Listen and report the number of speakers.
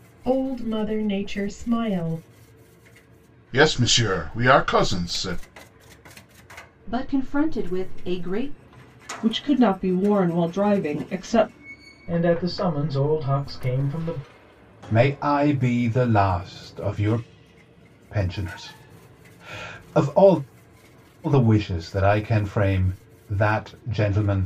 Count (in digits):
6